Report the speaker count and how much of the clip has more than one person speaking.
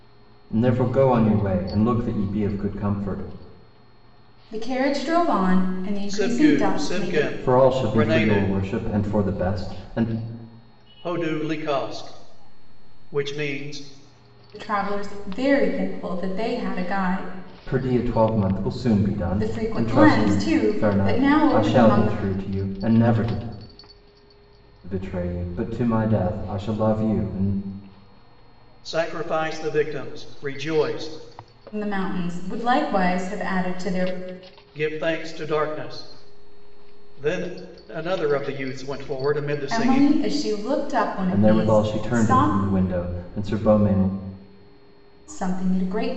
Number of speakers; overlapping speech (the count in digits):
3, about 14%